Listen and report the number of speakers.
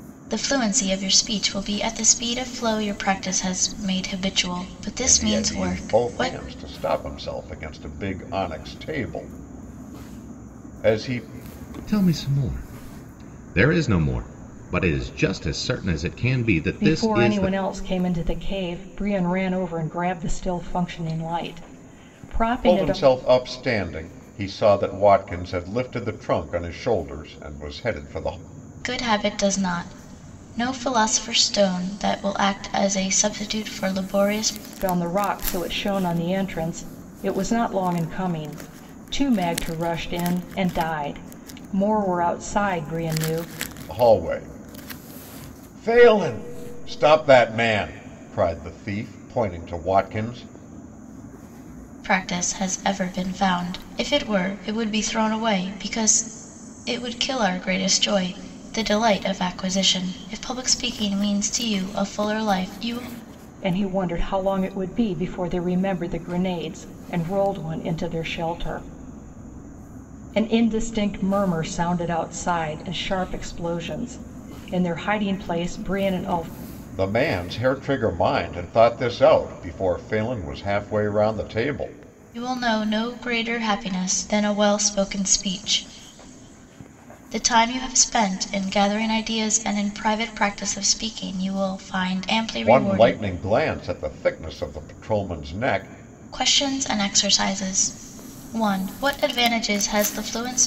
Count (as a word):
four